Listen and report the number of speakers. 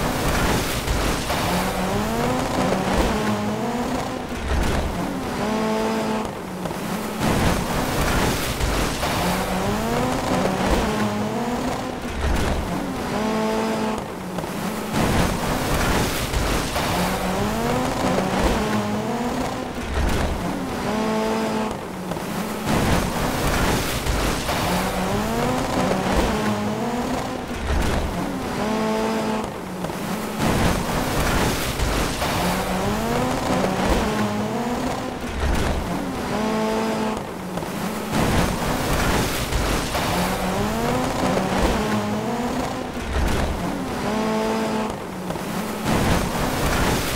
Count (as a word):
zero